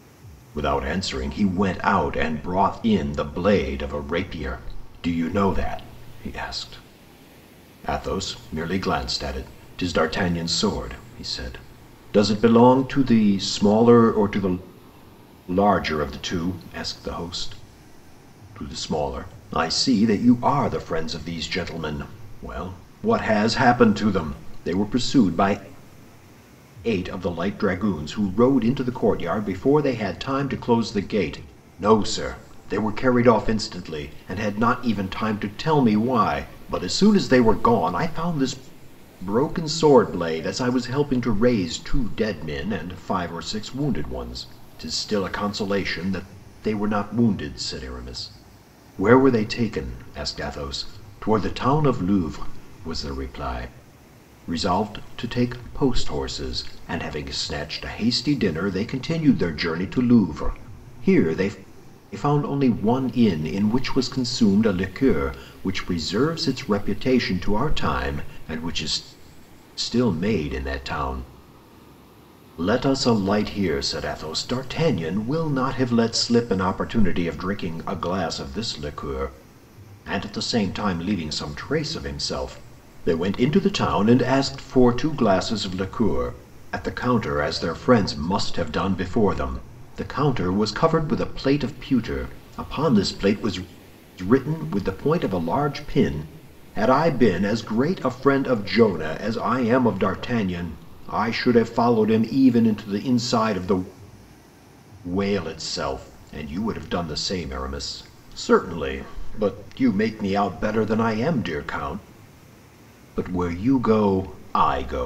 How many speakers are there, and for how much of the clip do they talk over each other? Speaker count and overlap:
one, no overlap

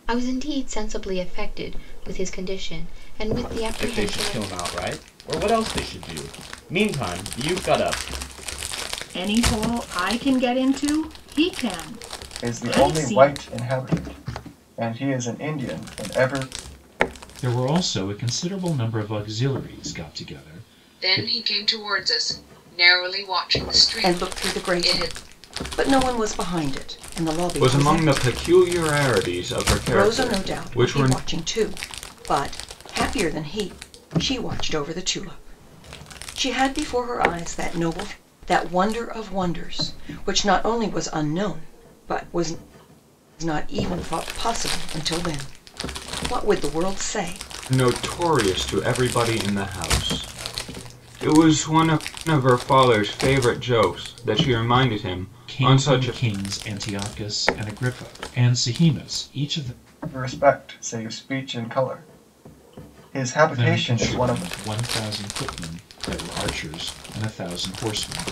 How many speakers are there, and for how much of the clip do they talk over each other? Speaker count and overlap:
eight, about 10%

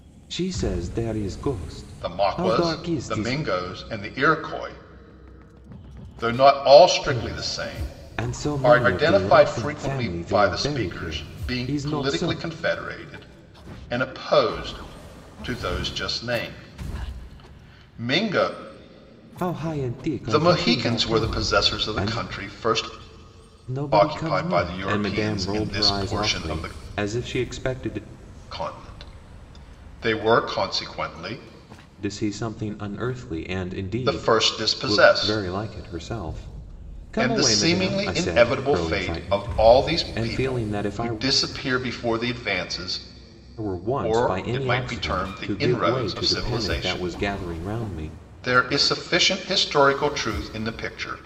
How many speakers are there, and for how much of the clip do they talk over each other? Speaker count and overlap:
two, about 40%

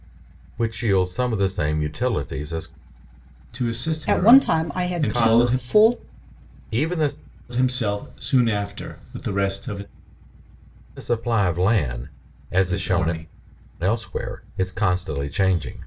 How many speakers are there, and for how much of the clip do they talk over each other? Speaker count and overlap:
three, about 16%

